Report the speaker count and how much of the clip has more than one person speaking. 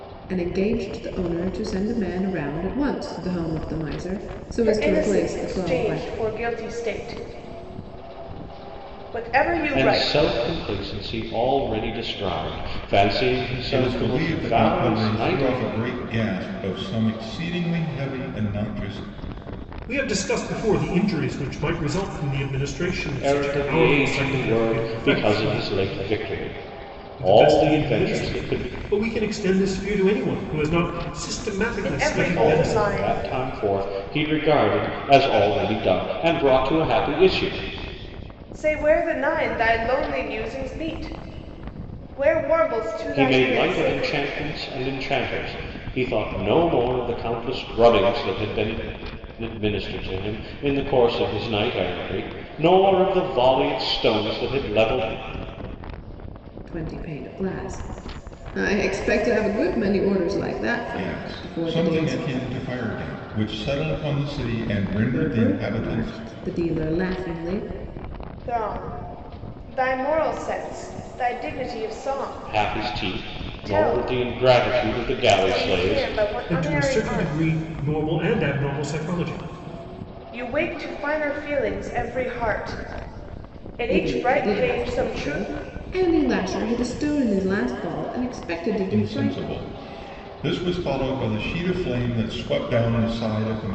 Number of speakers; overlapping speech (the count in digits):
5, about 20%